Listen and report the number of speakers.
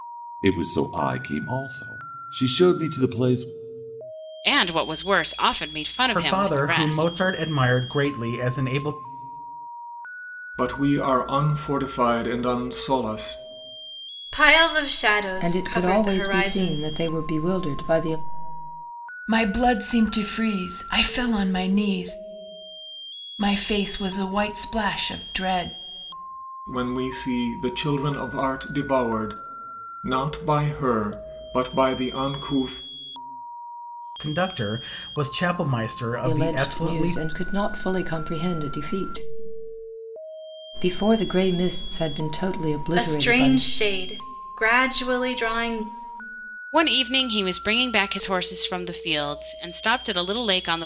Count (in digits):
7